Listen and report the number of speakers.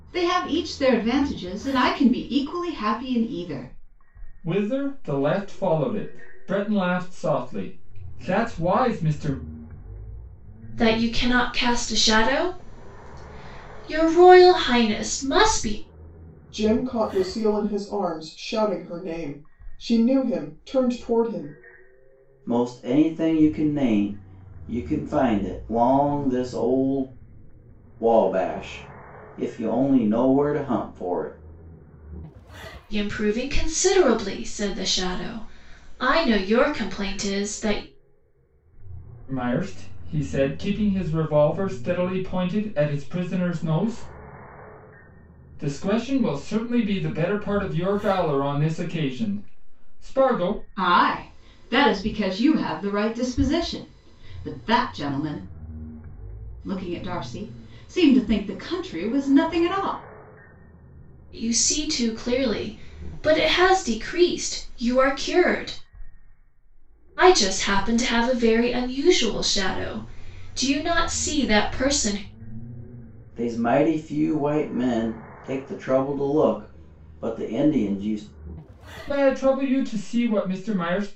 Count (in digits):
5